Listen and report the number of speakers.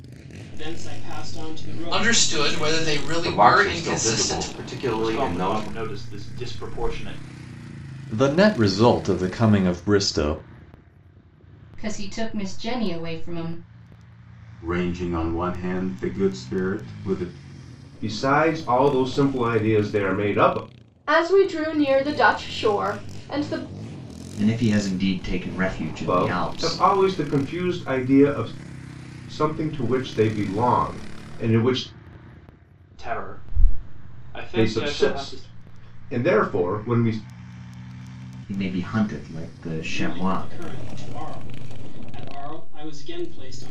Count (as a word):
ten